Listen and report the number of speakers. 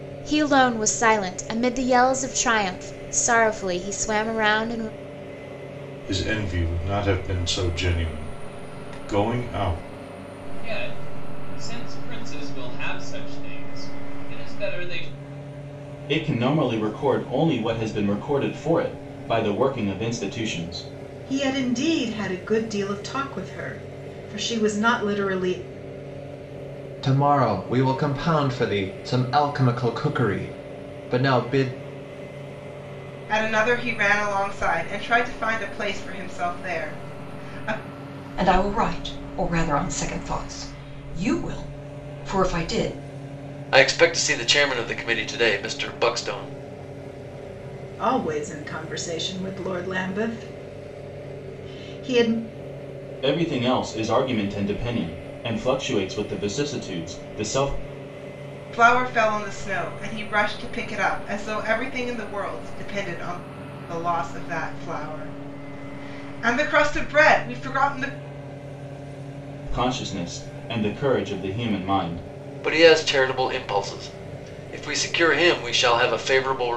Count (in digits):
9